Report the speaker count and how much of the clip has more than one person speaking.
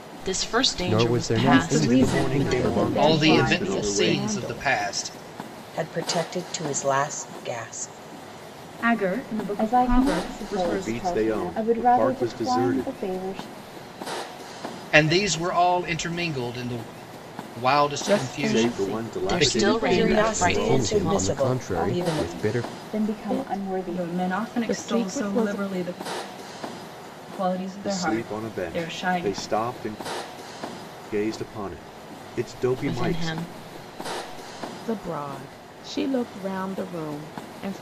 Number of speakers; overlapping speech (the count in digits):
9, about 43%